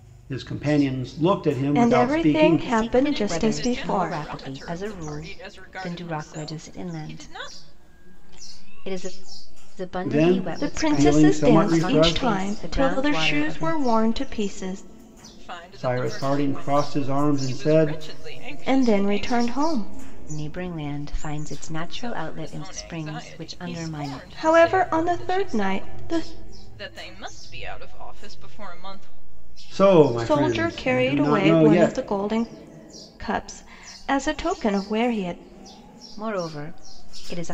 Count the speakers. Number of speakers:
four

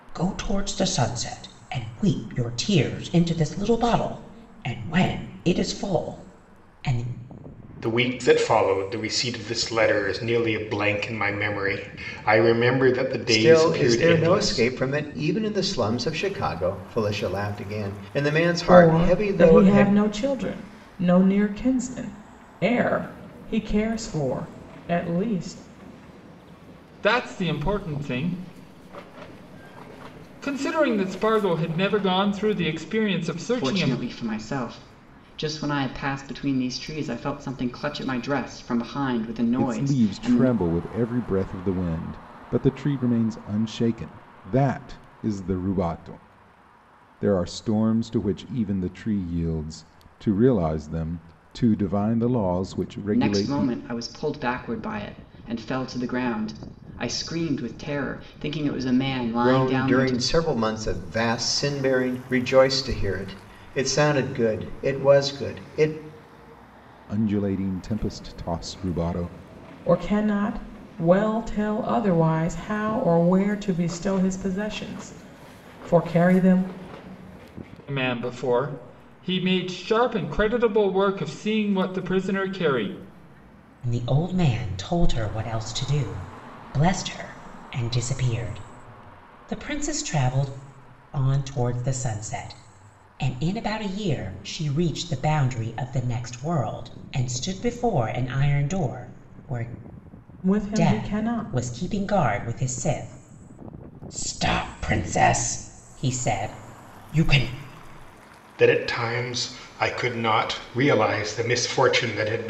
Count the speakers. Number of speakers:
seven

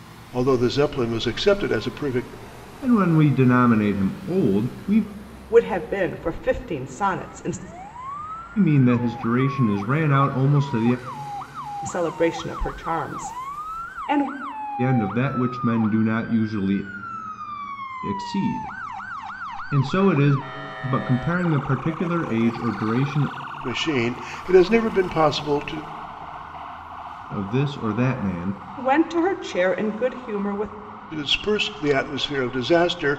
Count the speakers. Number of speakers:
three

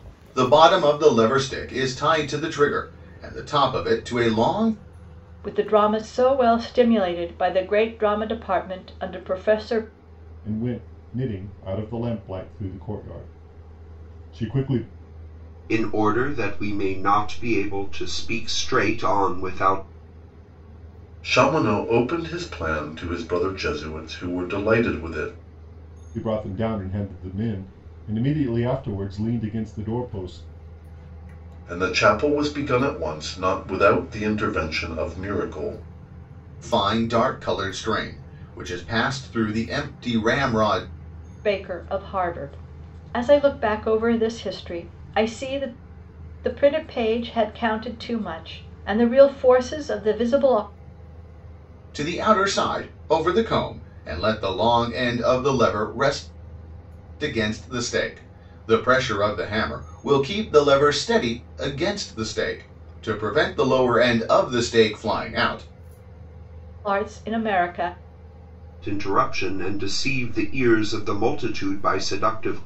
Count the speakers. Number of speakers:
five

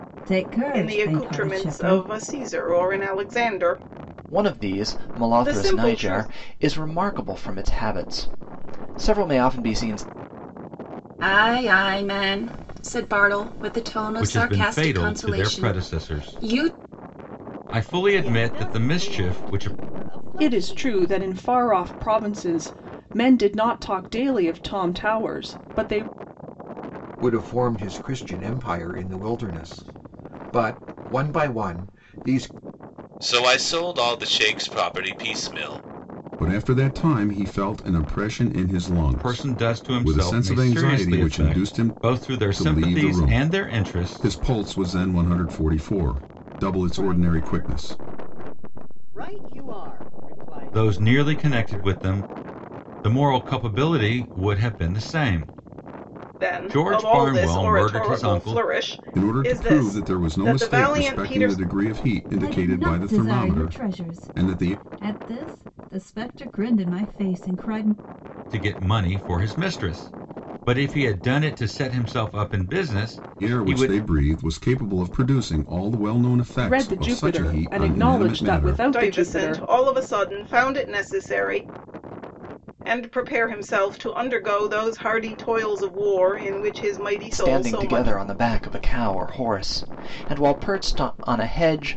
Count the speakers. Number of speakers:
ten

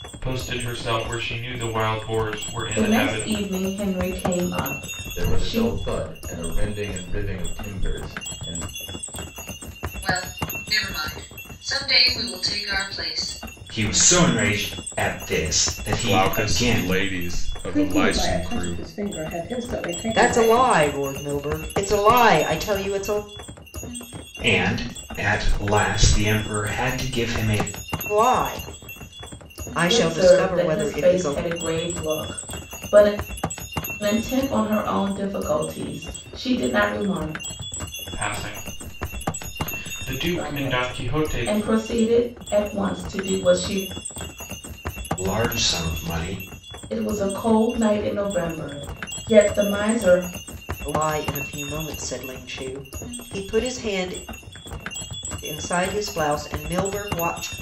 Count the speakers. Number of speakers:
eight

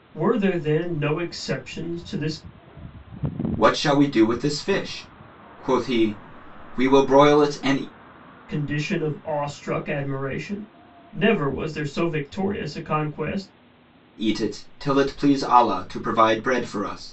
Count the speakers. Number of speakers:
two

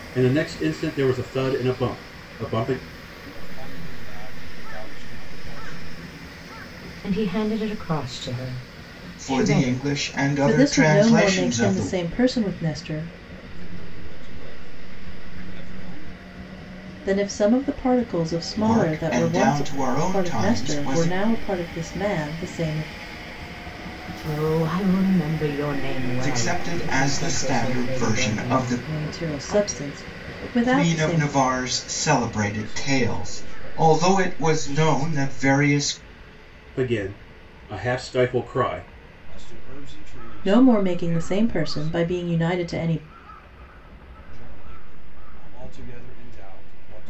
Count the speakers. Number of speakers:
five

